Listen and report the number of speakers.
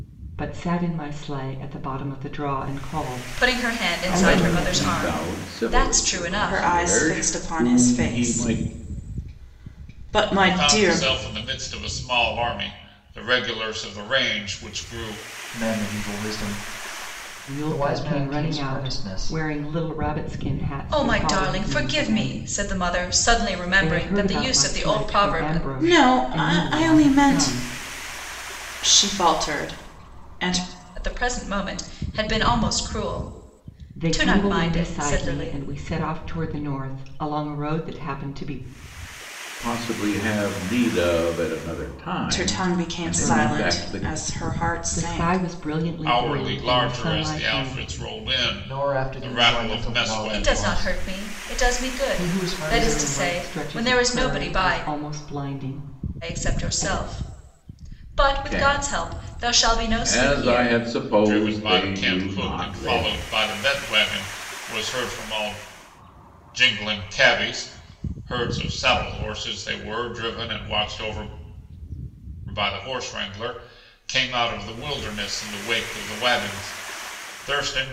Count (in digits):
6